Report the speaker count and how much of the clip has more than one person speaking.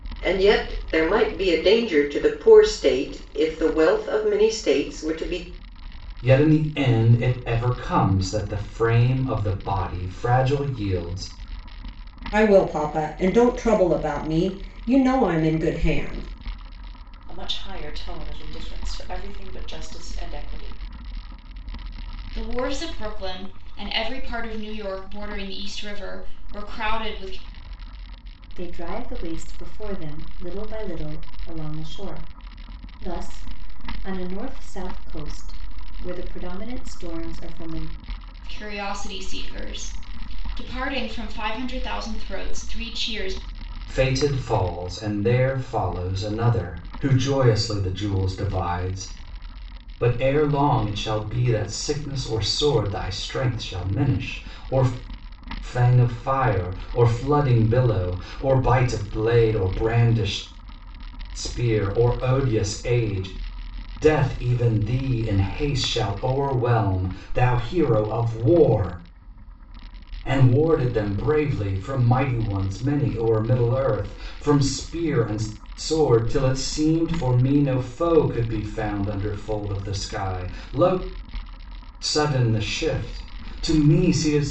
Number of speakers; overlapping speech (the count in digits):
6, no overlap